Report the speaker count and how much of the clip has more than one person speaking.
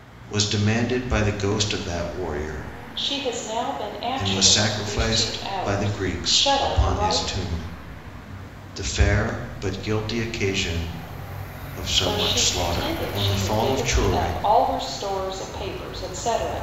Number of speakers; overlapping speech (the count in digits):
2, about 33%